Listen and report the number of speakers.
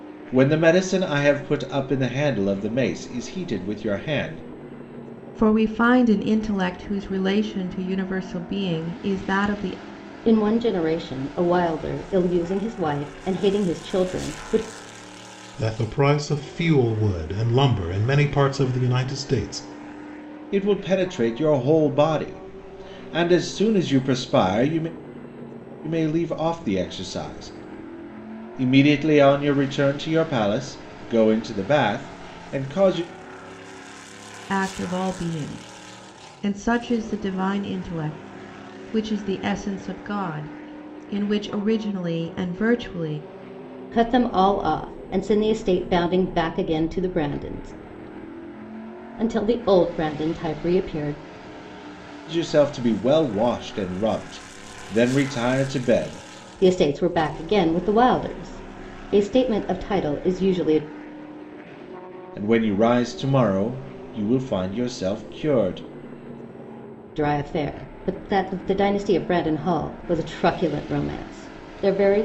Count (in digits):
4